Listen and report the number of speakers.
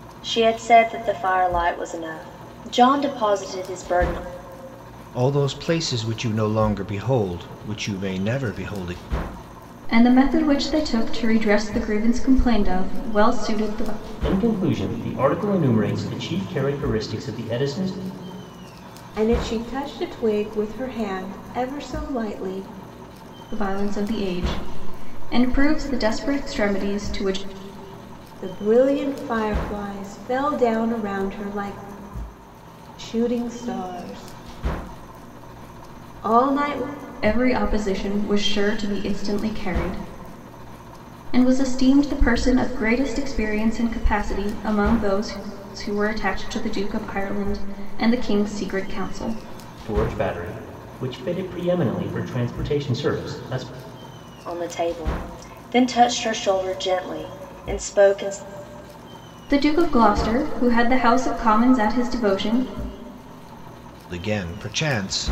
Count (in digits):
5